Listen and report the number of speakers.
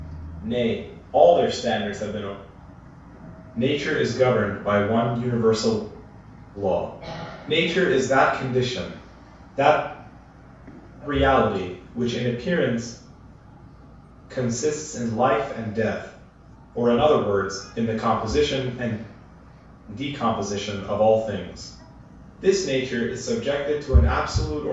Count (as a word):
one